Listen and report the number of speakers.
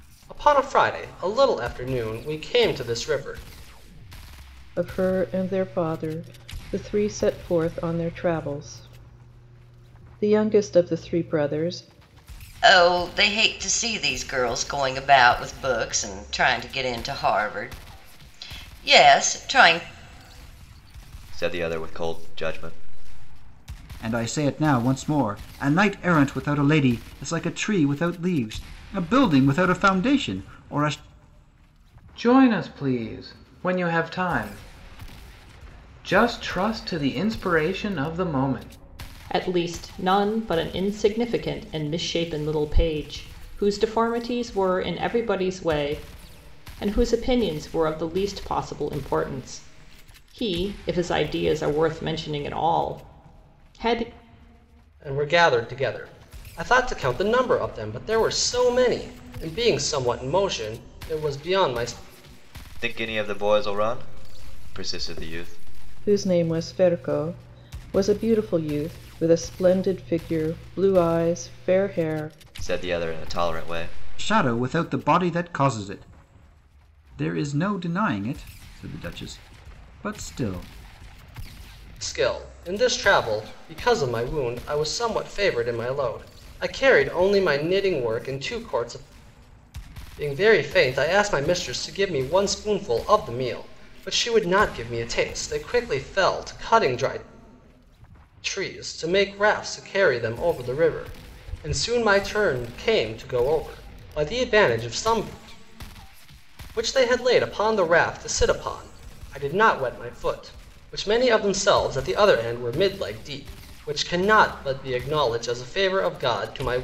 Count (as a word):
seven